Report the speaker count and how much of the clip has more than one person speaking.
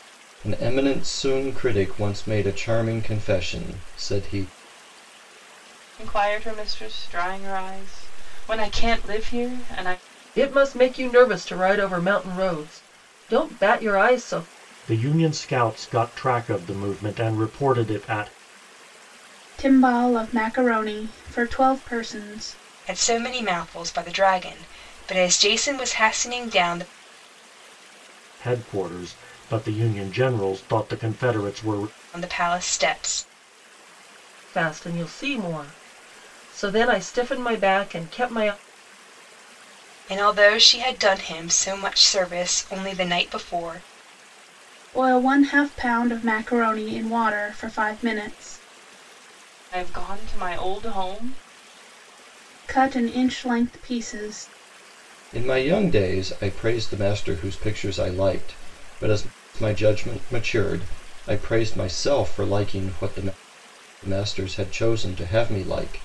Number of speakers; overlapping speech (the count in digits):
6, no overlap